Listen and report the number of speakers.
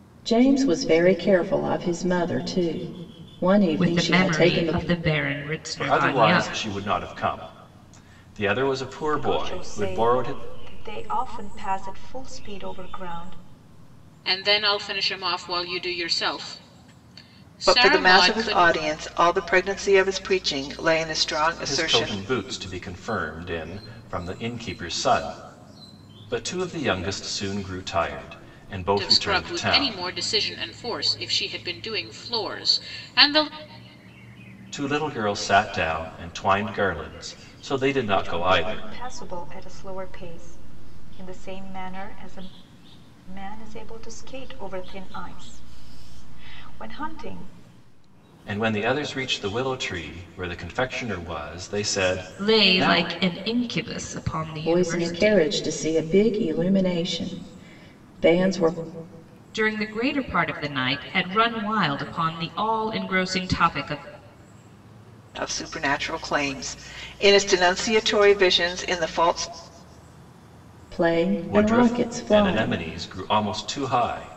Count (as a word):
six